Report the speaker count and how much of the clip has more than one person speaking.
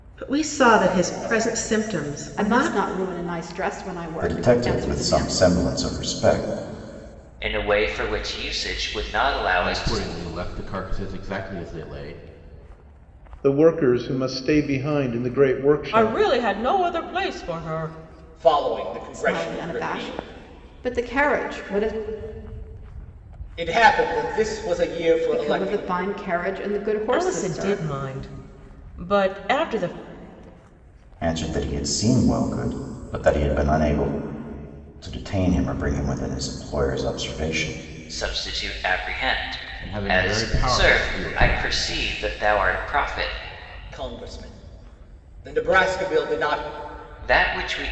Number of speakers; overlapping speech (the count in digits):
8, about 14%